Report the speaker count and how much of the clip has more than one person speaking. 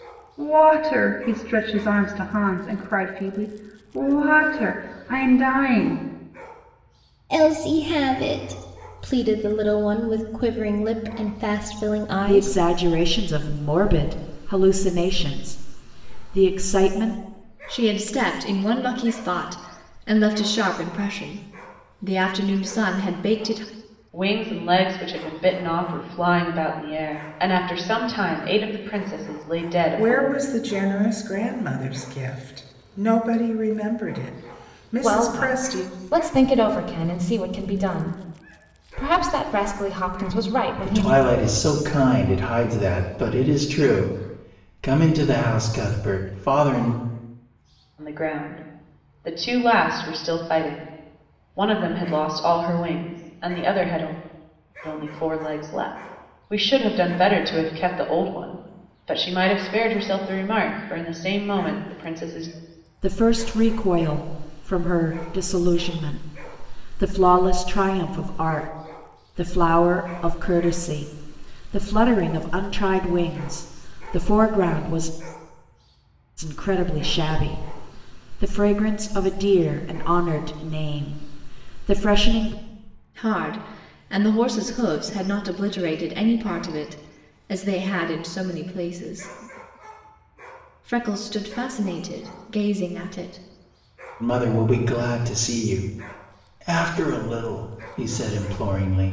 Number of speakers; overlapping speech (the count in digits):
8, about 2%